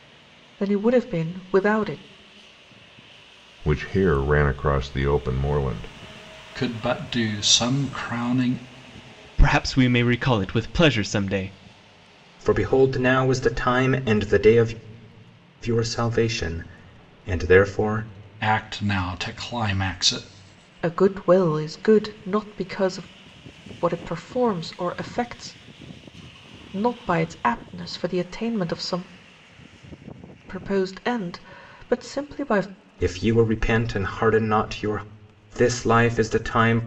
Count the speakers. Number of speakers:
5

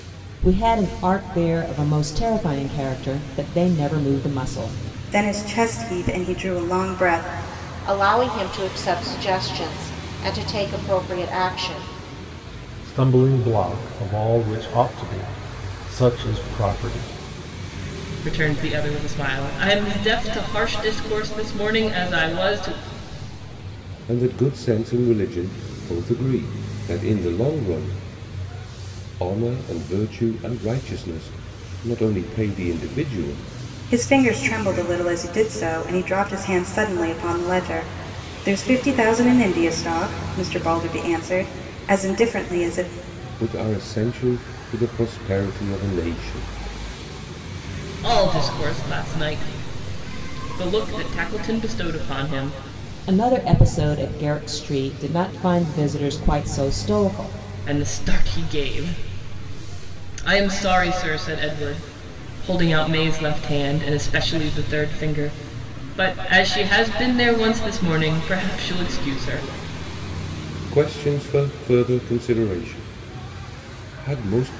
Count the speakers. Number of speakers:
6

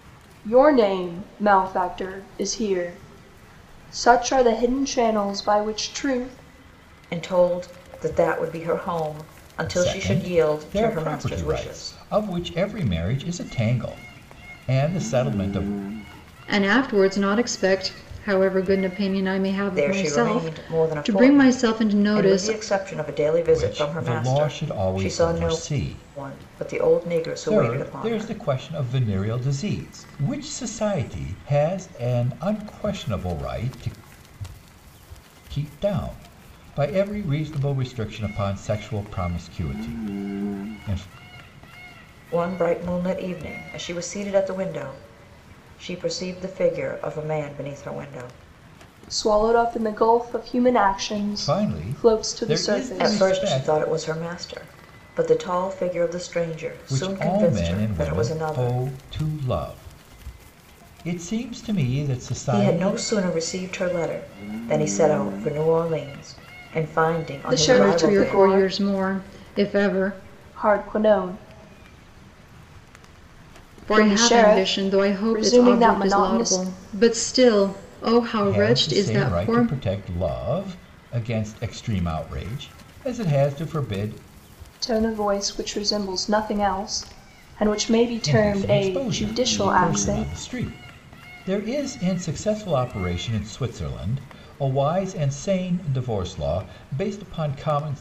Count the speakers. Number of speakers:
4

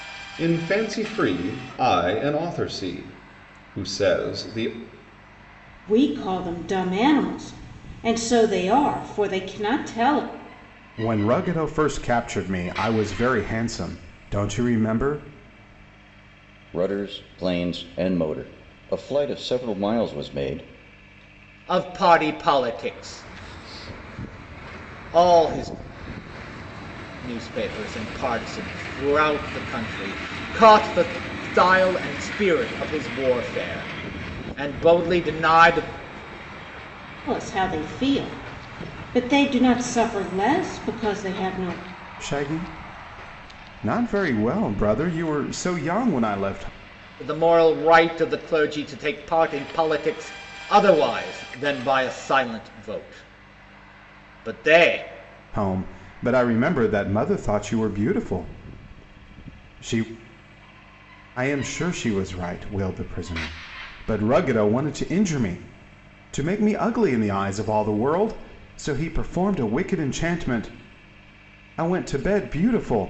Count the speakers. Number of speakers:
5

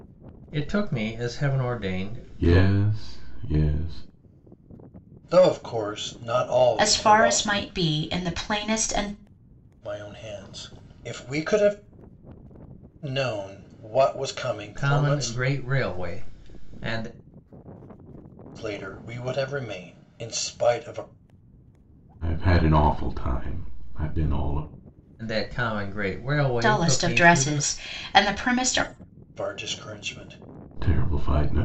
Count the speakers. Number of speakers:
4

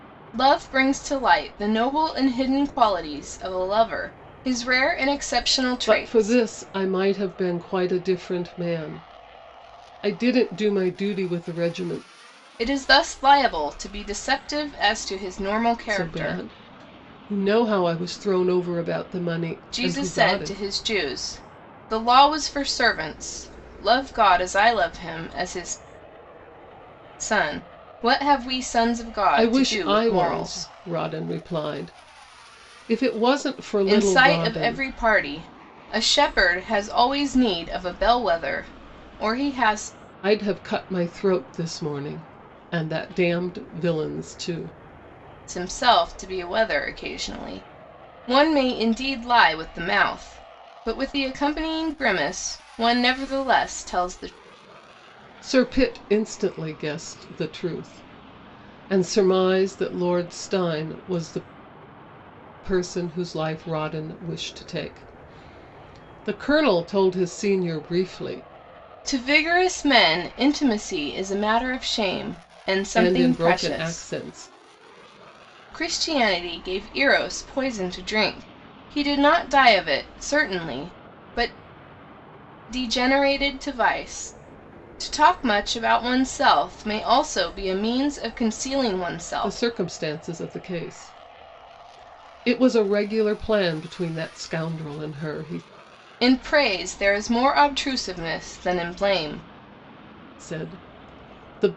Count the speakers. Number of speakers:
2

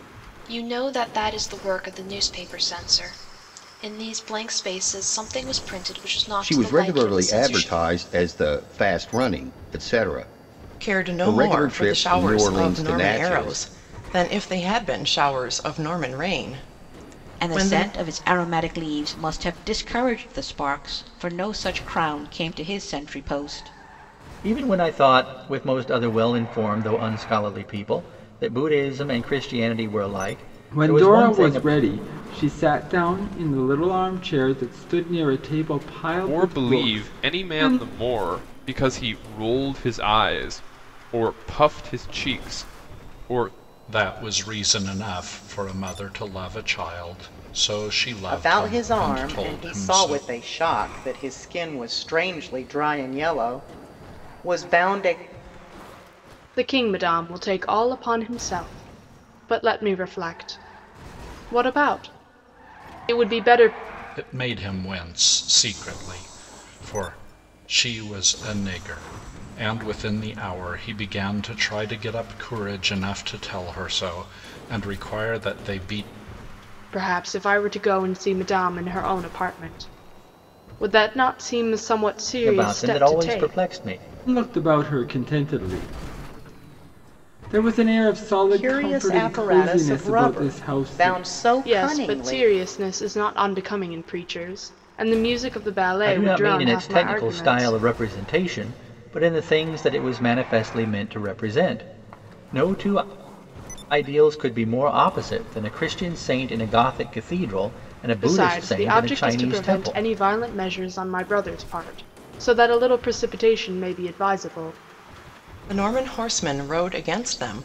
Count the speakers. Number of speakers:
10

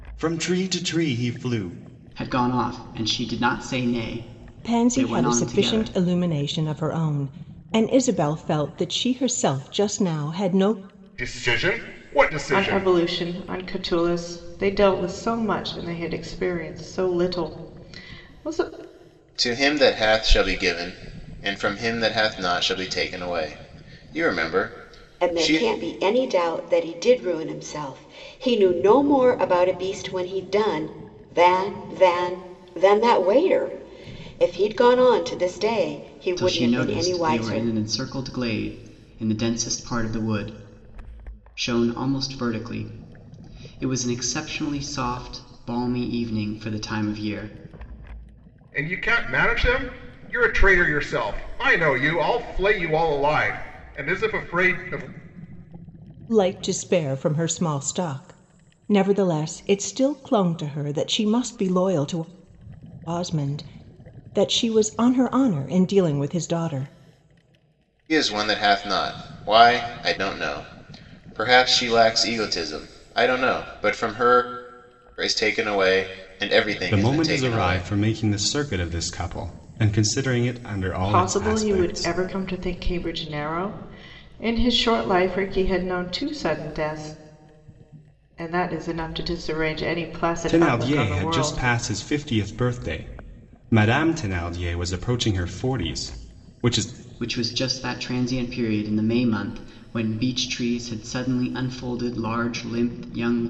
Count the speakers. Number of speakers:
7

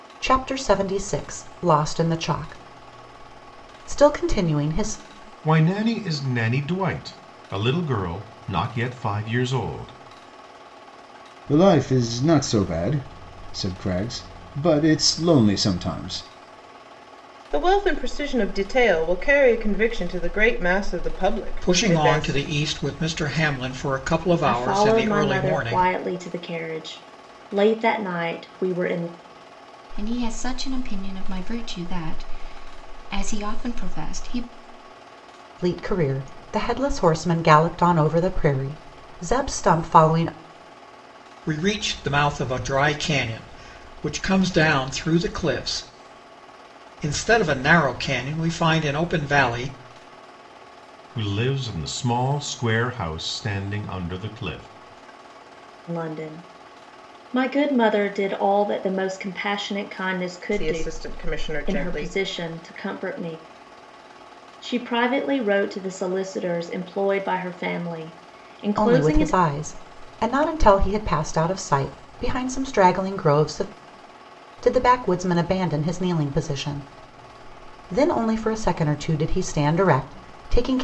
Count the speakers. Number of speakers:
7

